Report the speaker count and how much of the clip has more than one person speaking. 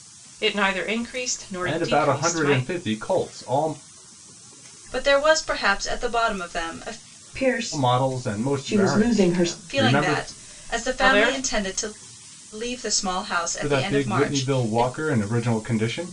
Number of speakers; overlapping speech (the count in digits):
4, about 38%